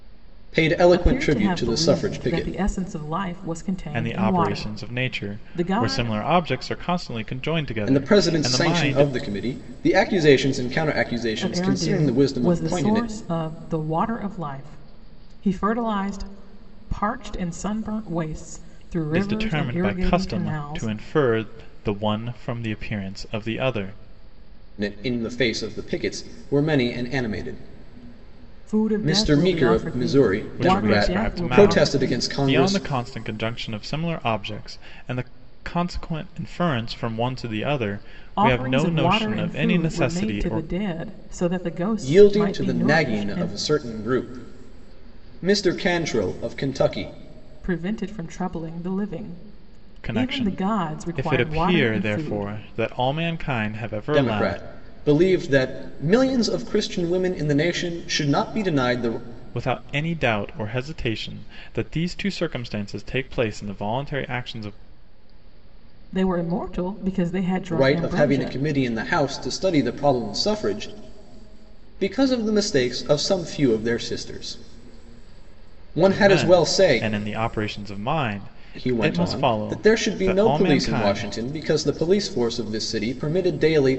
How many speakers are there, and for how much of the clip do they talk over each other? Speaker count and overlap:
three, about 29%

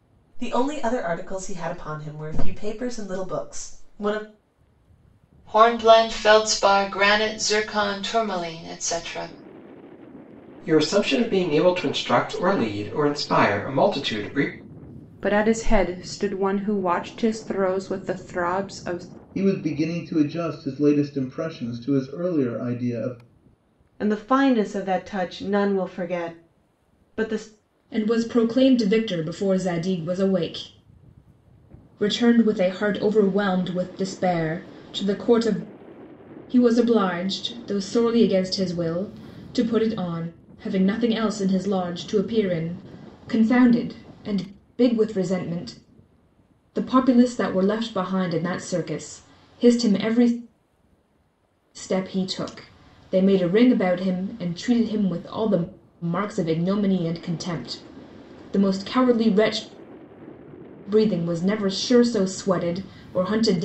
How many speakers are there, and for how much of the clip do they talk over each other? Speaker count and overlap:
seven, no overlap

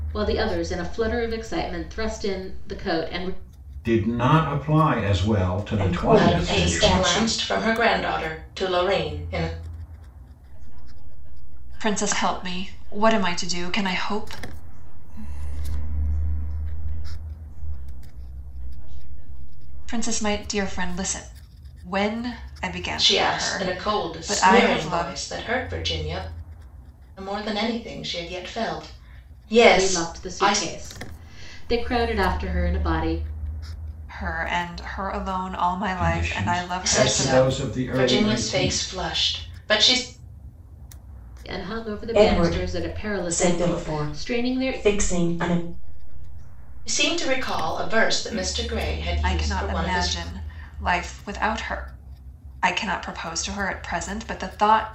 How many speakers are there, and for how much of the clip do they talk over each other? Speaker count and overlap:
six, about 32%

